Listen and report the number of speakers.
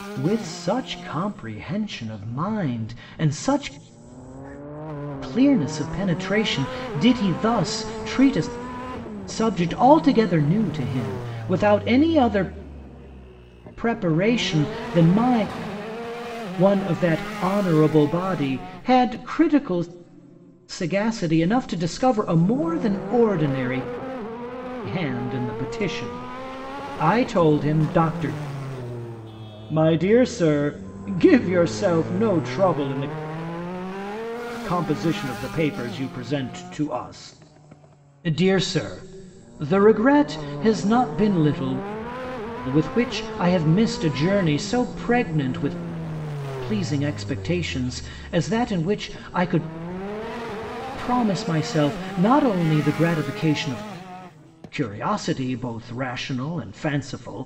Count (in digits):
1